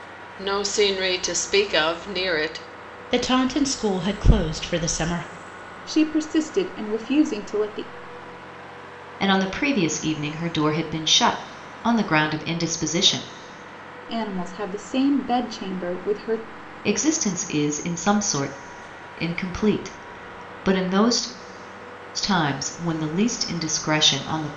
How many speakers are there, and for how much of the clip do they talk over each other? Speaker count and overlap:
four, no overlap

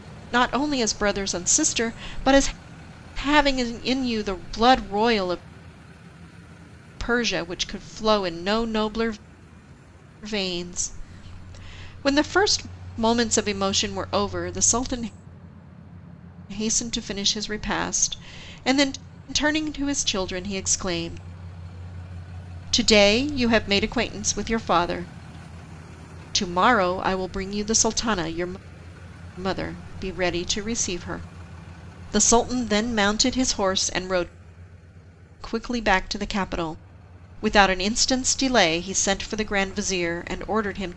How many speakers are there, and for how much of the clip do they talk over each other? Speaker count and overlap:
one, no overlap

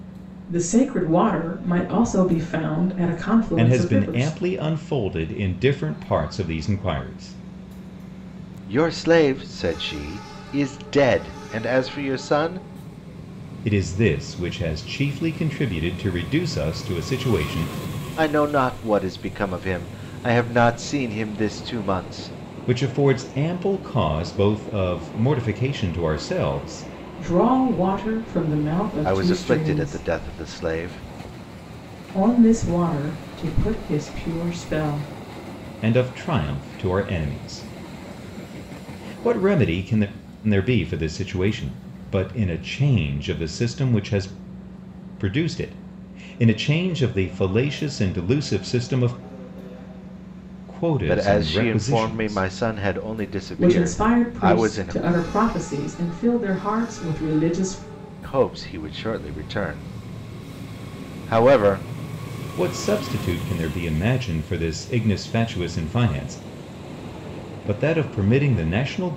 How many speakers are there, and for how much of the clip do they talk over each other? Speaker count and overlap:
three, about 7%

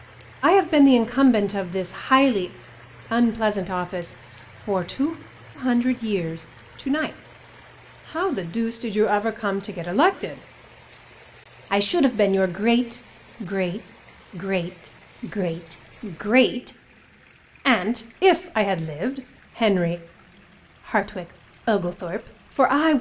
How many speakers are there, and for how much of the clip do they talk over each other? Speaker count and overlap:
one, no overlap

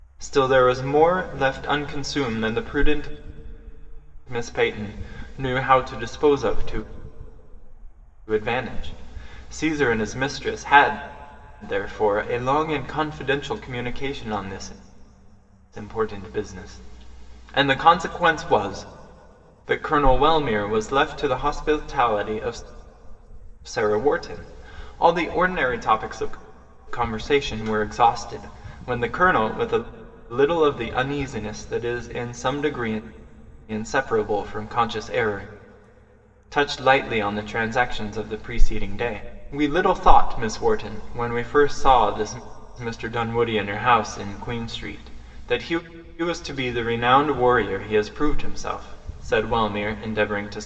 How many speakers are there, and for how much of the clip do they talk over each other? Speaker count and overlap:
one, no overlap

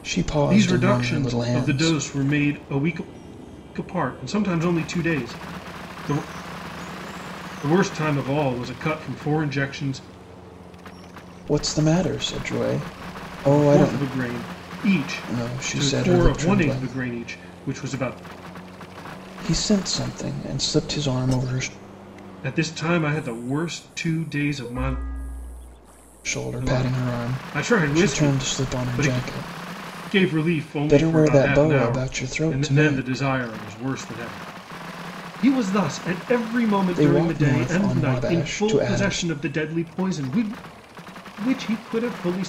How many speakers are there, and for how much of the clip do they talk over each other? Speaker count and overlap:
two, about 25%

